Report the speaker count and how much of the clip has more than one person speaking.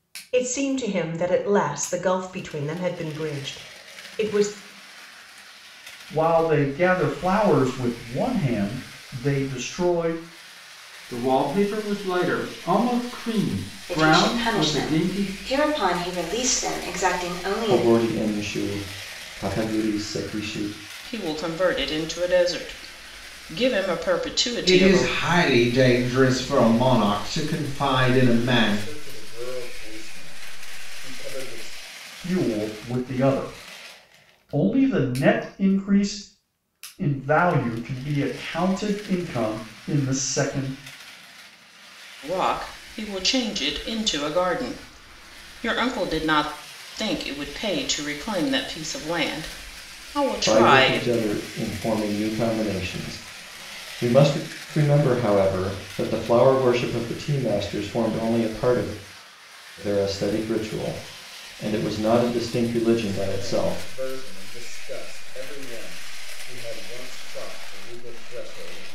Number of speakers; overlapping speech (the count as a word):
eight, about 7%